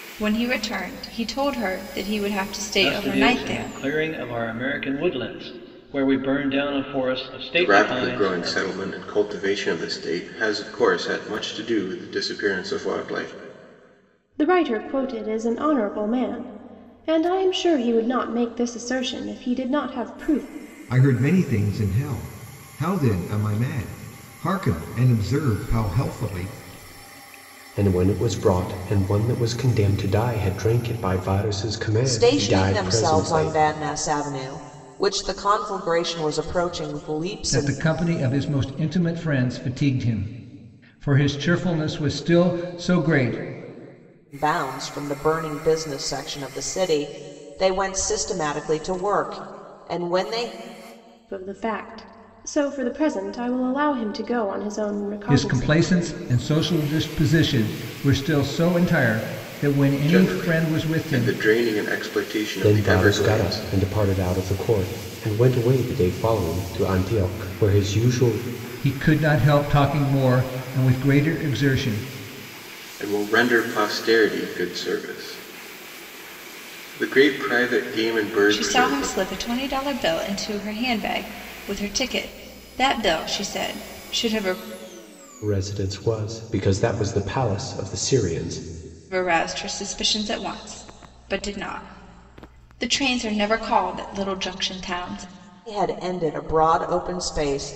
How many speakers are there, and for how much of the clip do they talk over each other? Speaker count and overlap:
8, about 8%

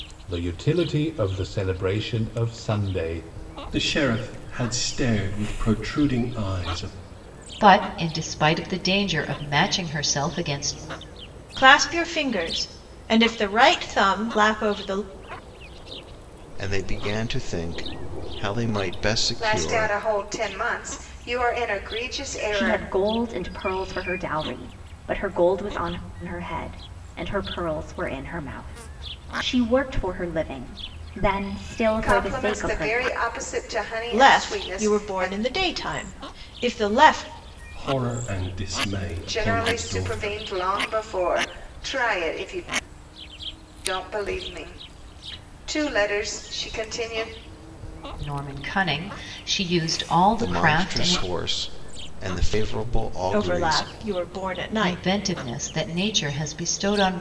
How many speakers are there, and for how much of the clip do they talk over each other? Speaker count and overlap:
7, about 11%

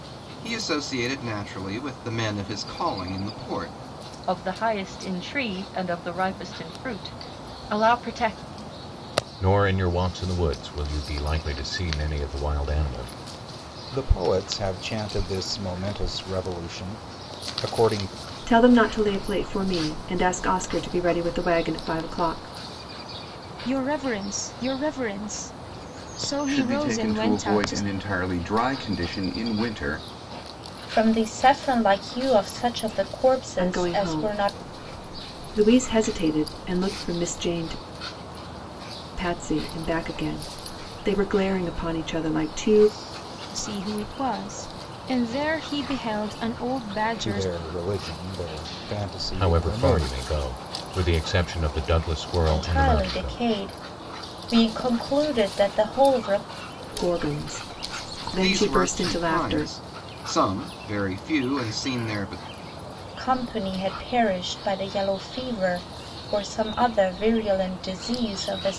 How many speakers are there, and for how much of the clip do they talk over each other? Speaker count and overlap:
8, about 9%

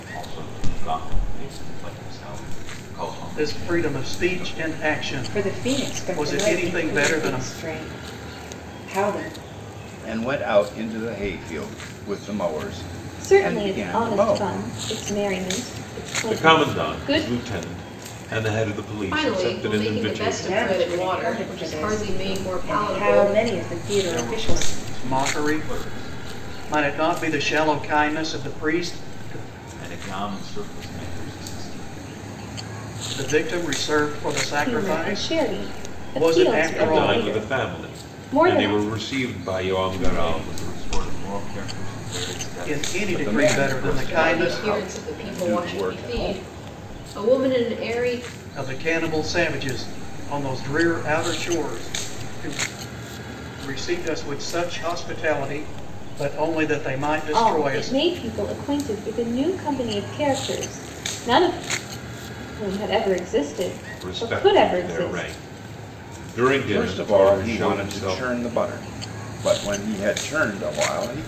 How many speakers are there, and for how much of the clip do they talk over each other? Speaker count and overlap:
7, about 35%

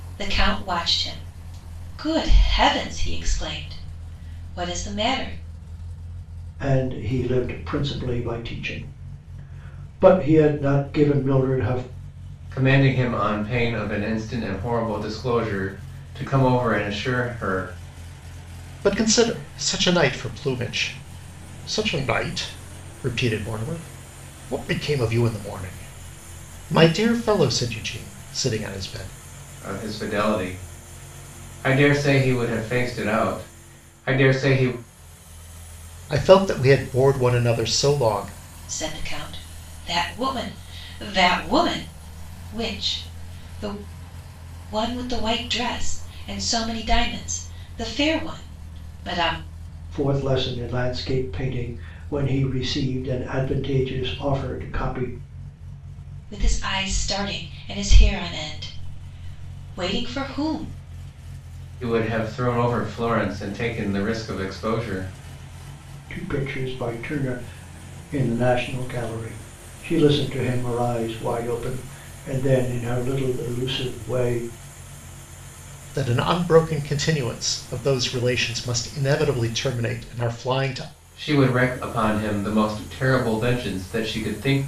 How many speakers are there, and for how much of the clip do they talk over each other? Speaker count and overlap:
4, no overlap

